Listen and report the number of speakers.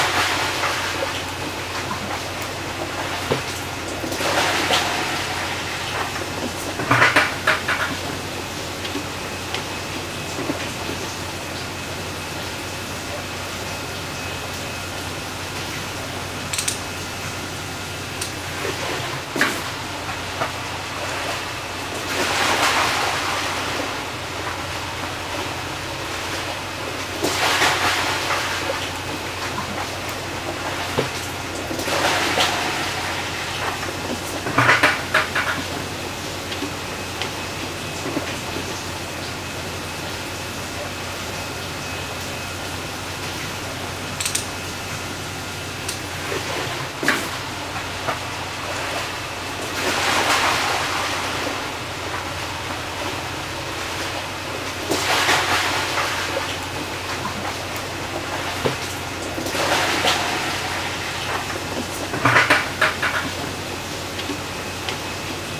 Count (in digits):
0